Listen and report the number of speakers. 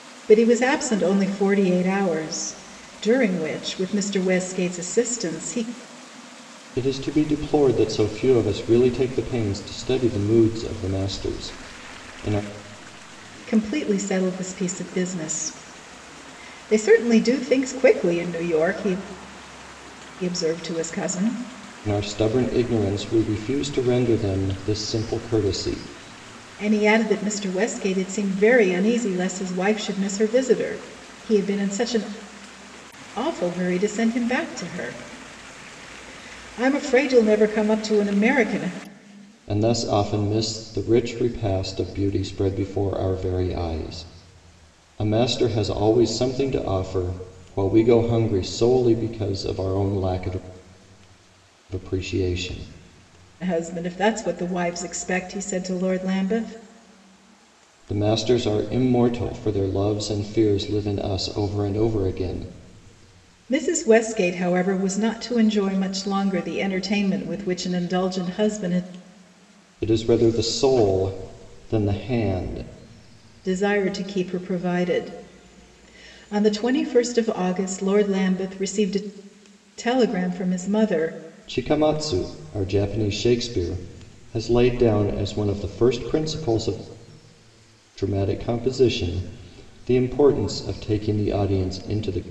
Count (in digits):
2